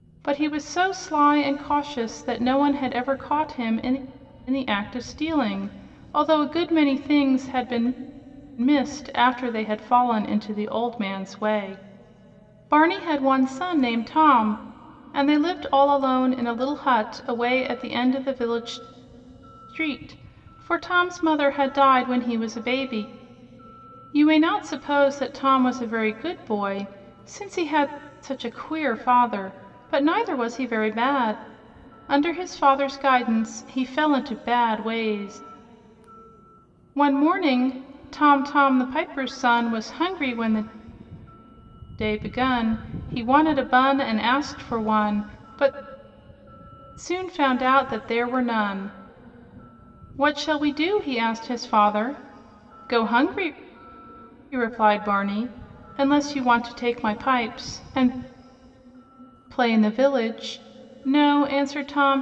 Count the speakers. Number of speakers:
one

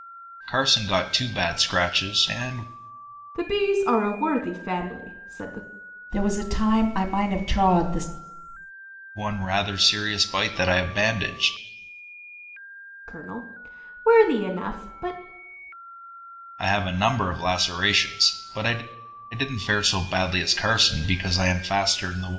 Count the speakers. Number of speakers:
three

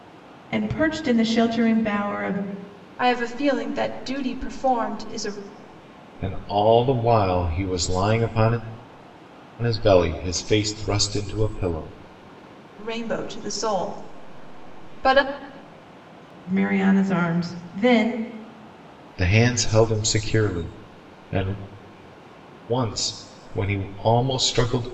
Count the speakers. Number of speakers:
three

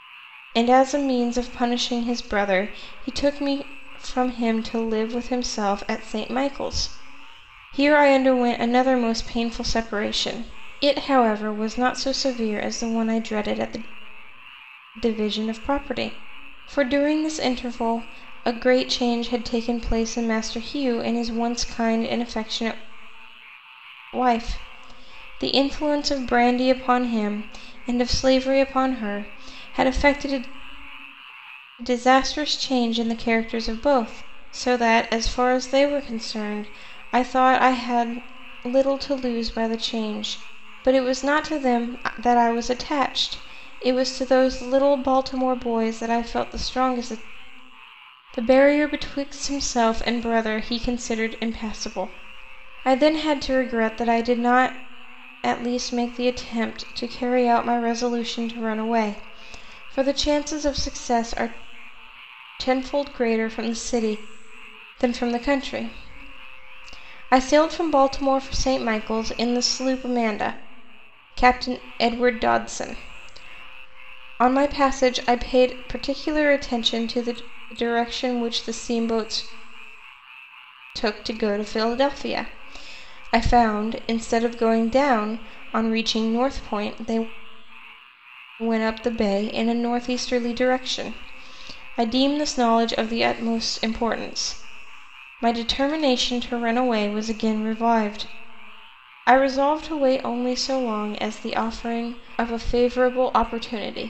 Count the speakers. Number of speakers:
one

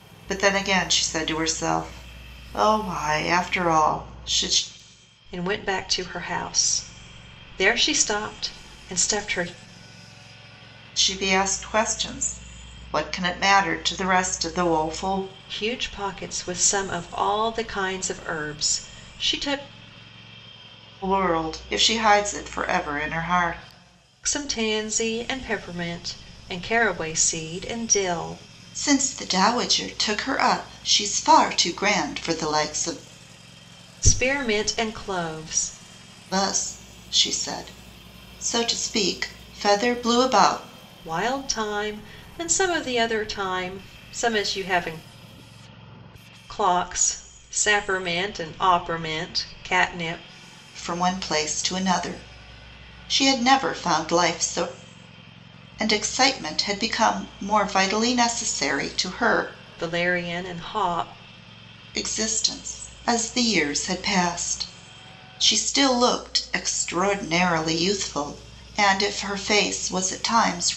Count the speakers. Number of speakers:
two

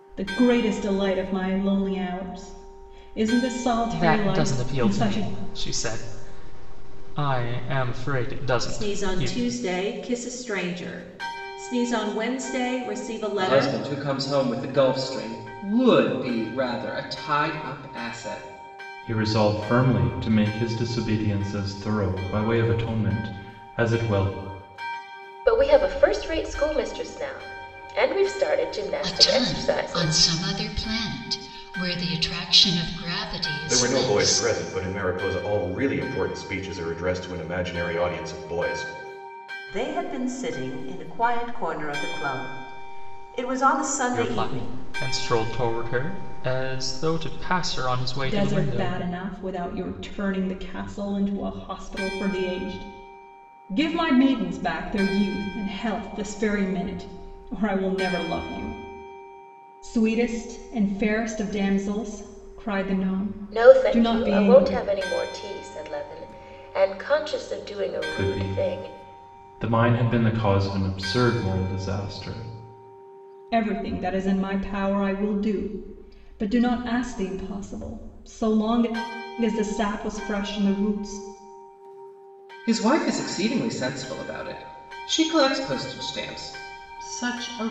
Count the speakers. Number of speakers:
nine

